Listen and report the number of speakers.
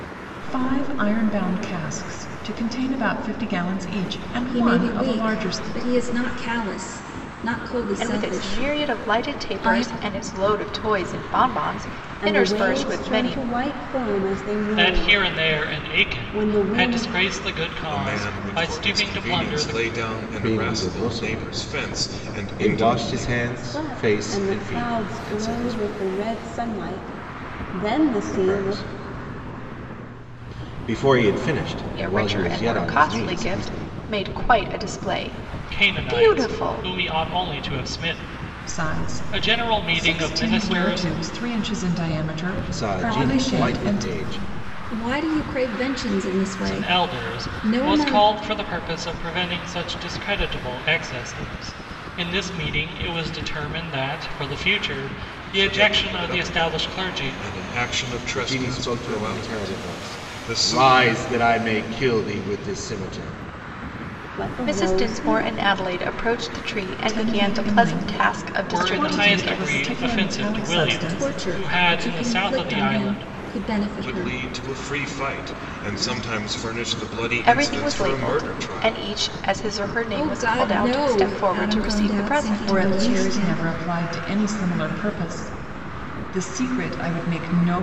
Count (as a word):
seven